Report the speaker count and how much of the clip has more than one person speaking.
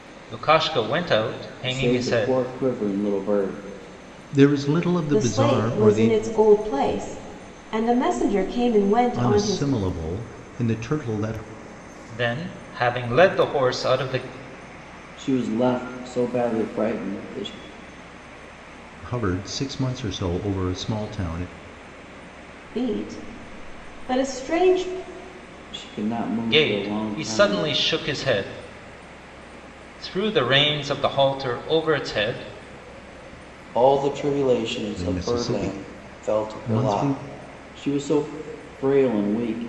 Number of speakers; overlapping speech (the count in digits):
4, about 14%